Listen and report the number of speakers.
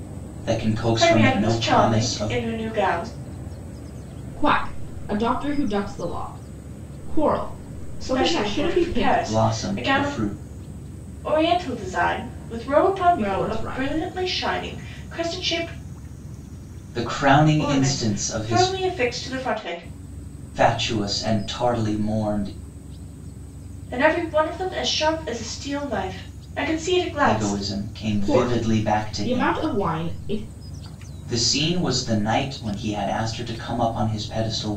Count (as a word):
three